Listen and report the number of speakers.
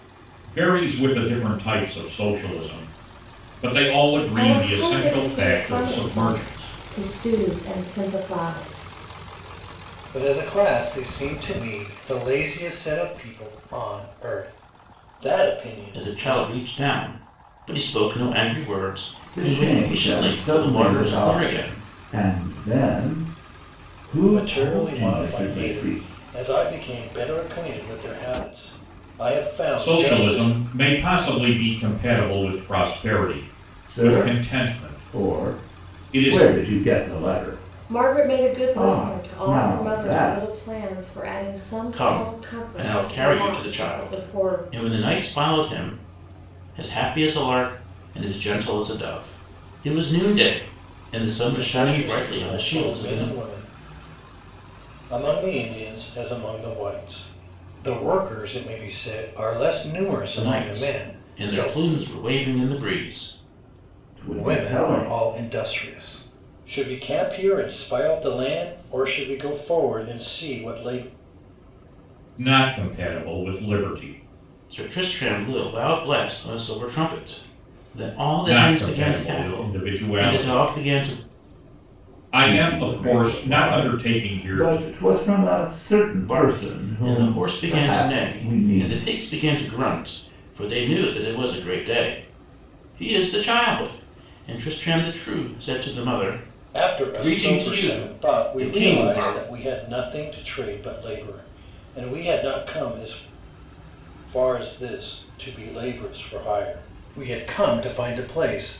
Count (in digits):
5